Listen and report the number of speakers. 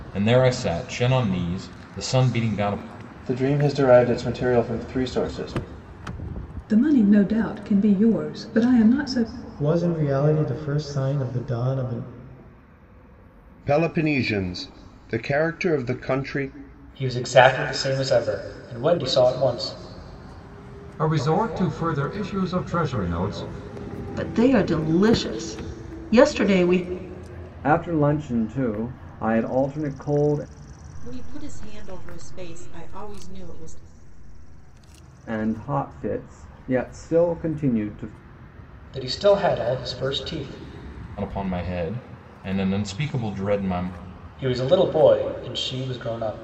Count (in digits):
10